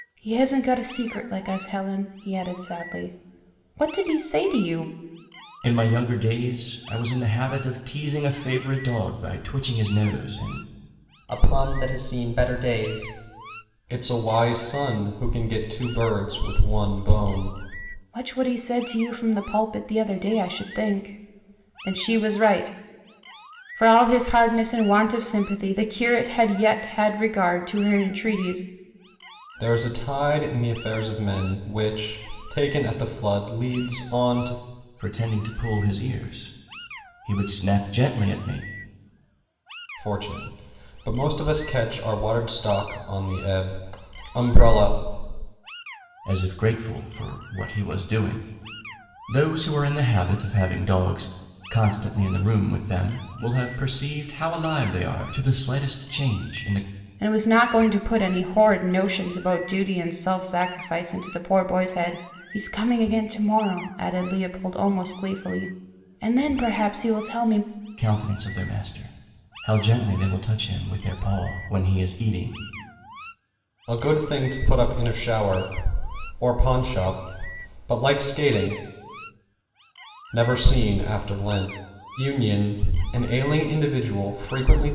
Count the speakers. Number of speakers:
three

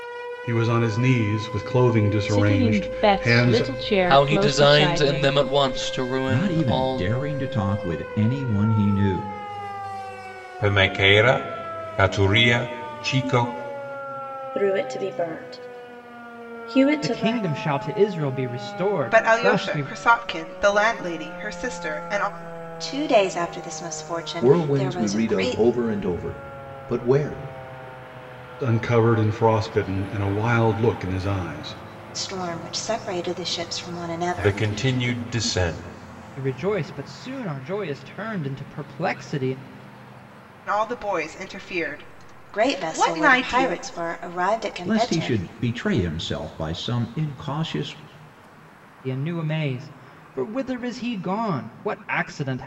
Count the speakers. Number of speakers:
ten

